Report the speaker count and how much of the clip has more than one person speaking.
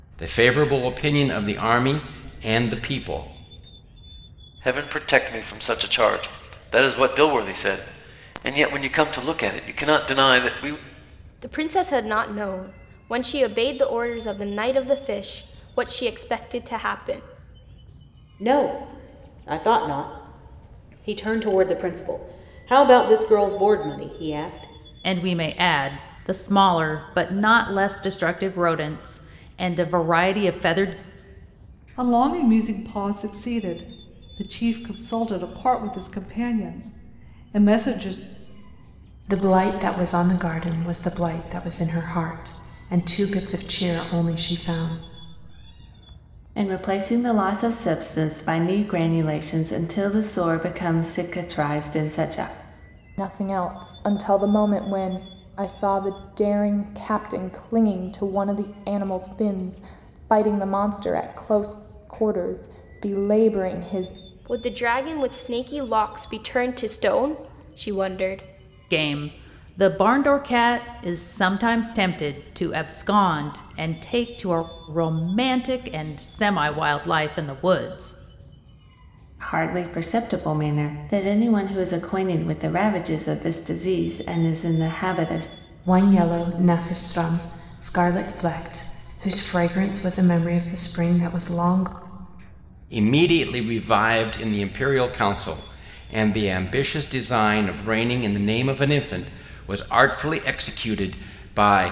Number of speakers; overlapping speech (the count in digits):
9, no overlap